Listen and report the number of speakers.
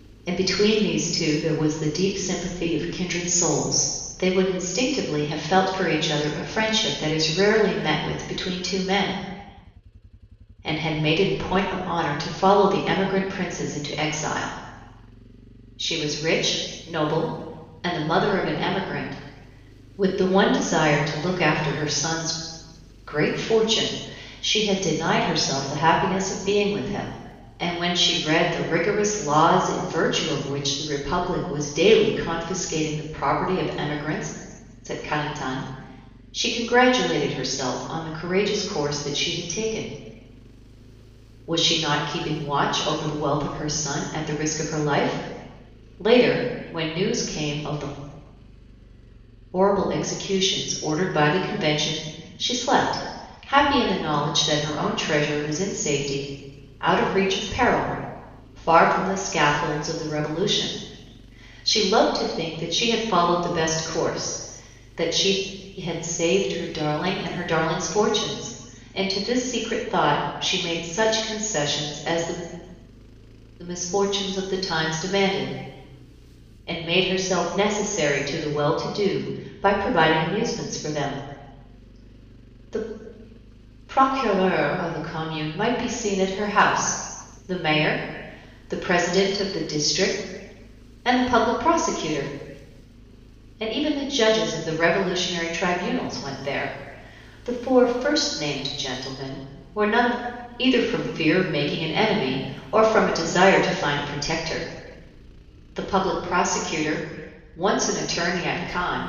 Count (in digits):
1